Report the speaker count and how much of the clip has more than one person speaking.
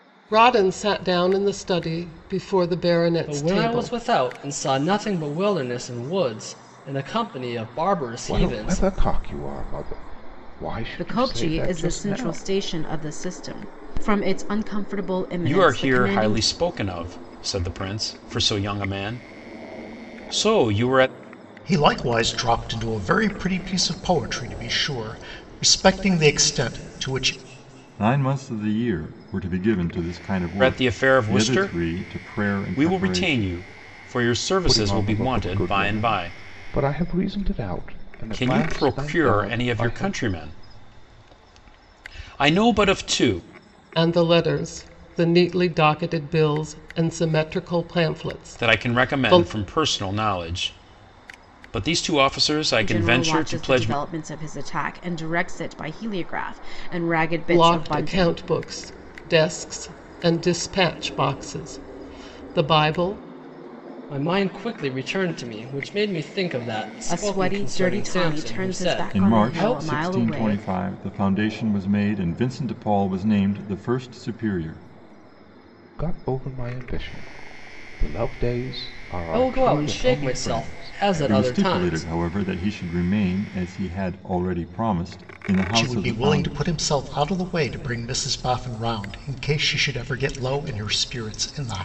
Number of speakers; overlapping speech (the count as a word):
seven, about 23%